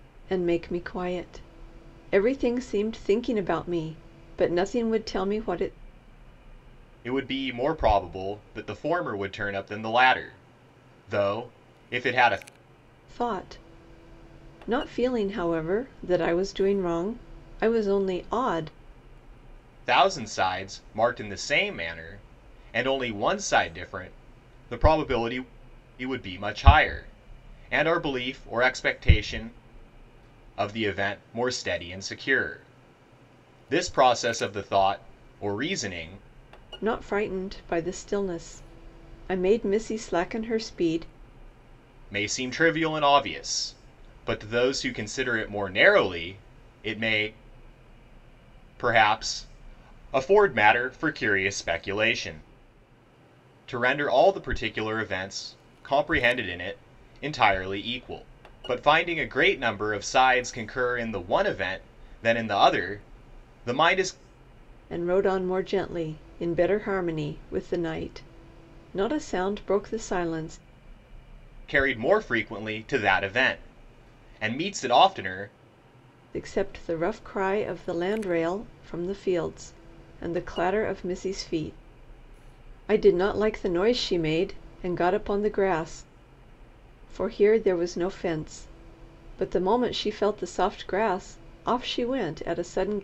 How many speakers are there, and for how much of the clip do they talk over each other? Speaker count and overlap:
two, no overlap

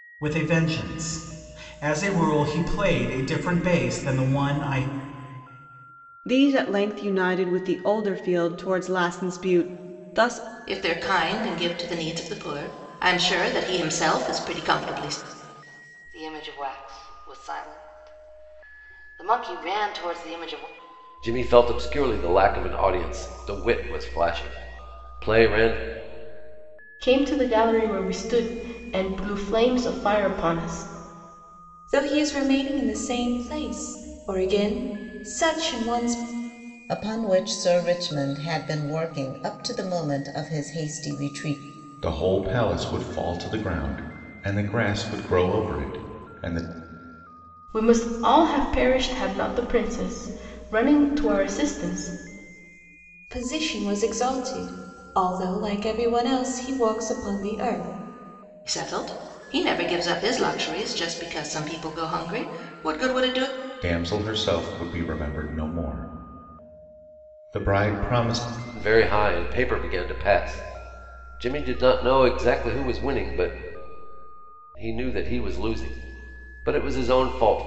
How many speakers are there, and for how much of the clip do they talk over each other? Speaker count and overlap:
nine, no overlap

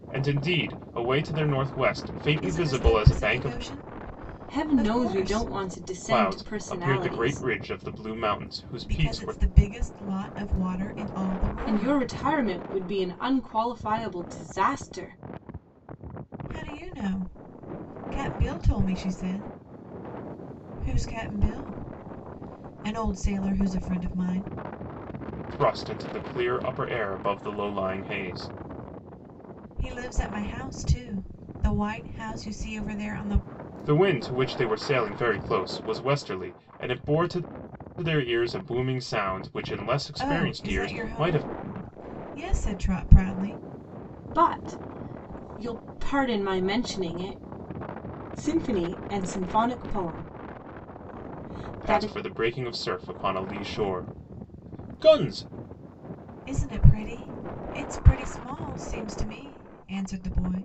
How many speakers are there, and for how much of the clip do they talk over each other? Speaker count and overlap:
three, about 11%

